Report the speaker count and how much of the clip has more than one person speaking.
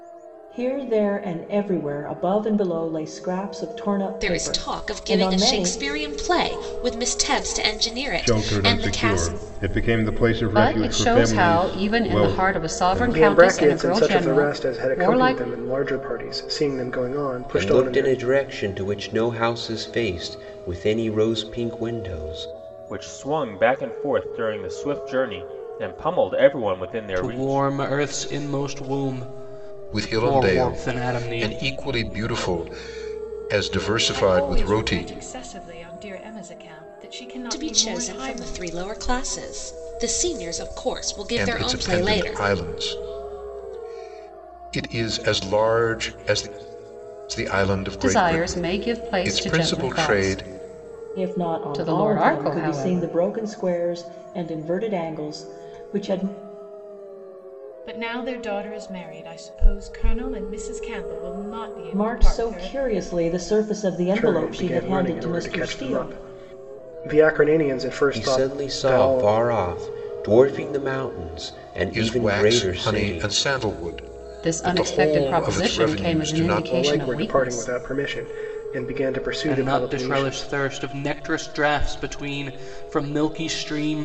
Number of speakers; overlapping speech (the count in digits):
10, about 34%